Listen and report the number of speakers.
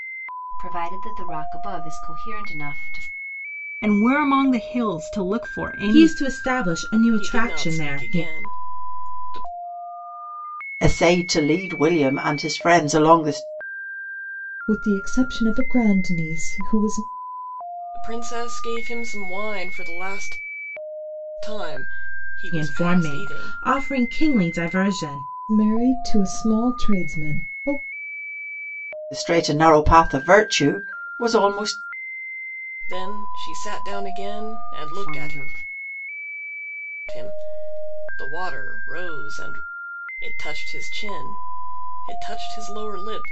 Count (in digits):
6